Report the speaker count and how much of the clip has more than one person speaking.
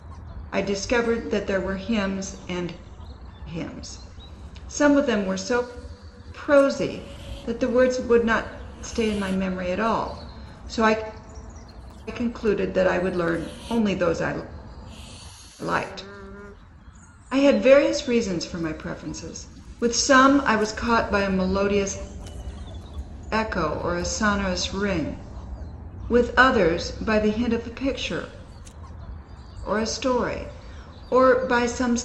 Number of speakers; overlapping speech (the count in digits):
1, no overlap